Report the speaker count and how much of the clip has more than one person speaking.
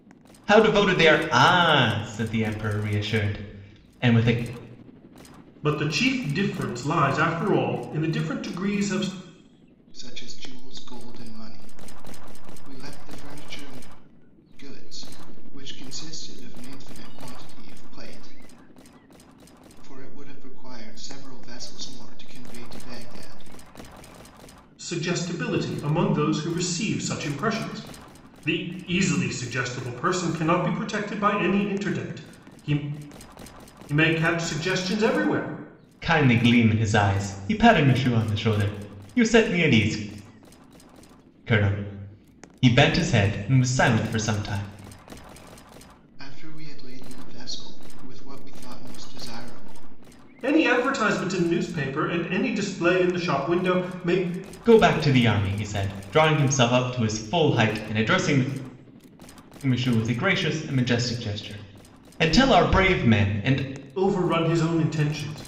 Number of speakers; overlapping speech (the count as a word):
three, no overlap